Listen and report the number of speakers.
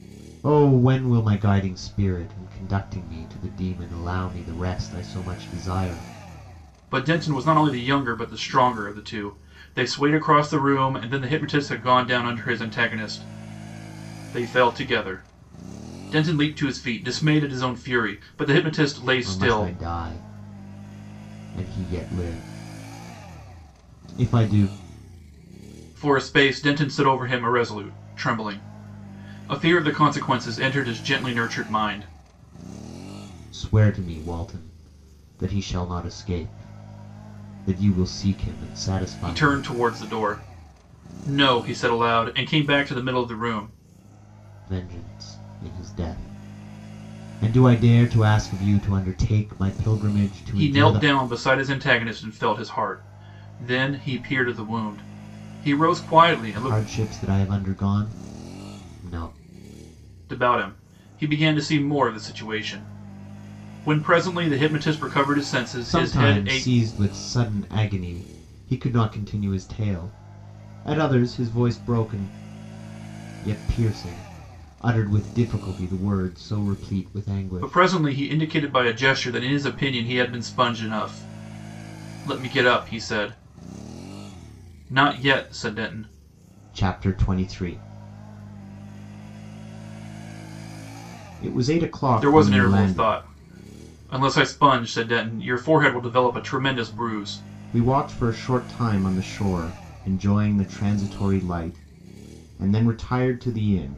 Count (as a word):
two